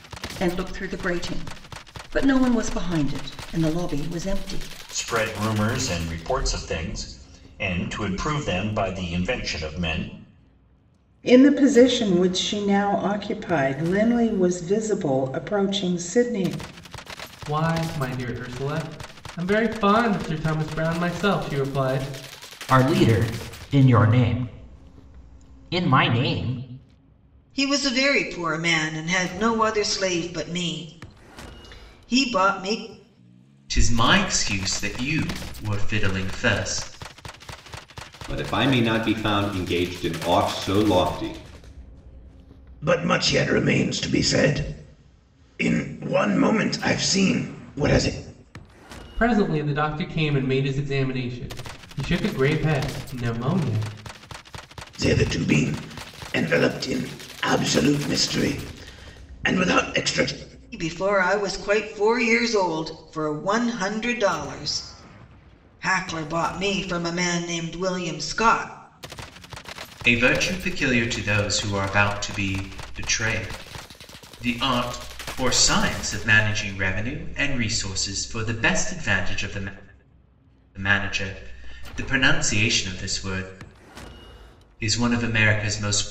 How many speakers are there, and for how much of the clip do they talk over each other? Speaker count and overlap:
nine, no overlap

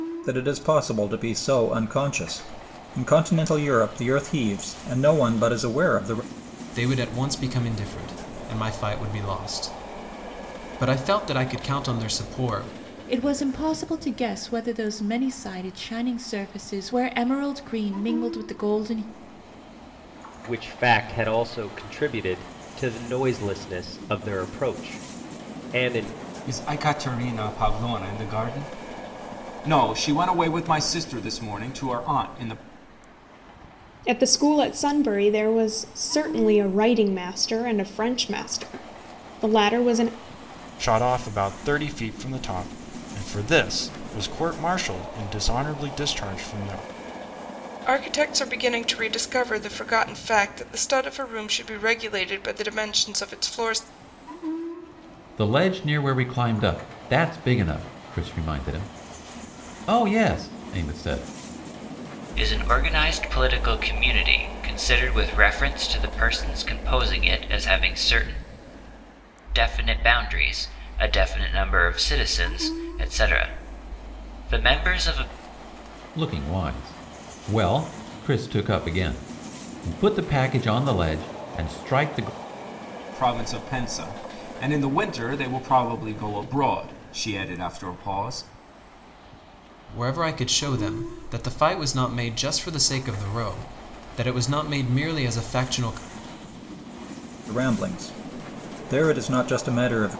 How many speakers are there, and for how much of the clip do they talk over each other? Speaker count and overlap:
ten, no overlap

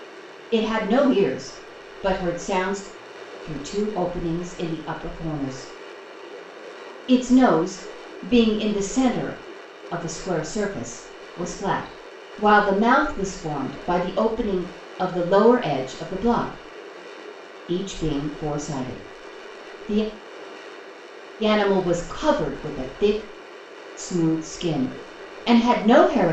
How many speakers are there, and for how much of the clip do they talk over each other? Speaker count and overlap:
one, no overlap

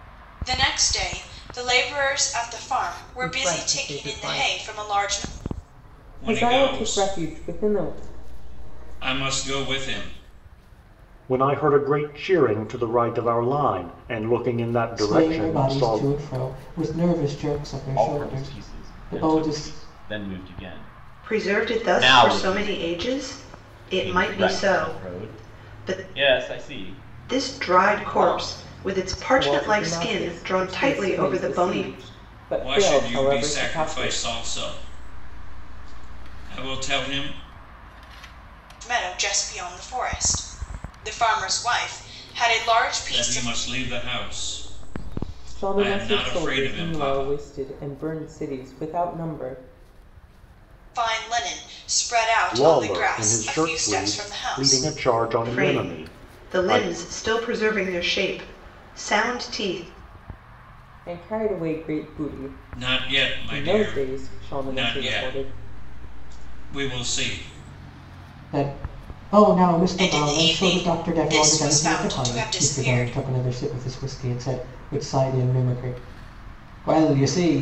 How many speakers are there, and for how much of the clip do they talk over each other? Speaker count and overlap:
seven, about 36%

